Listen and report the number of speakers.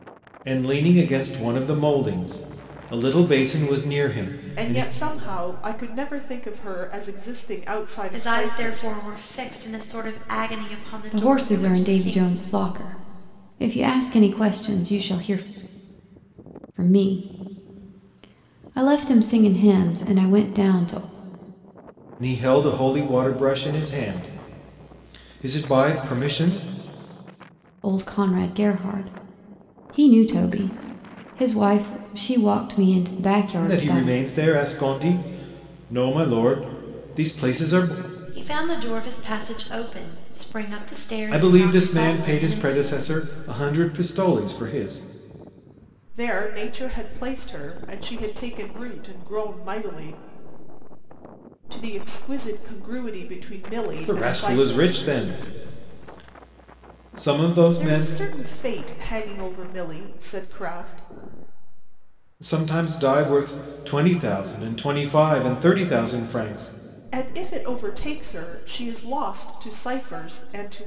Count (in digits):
4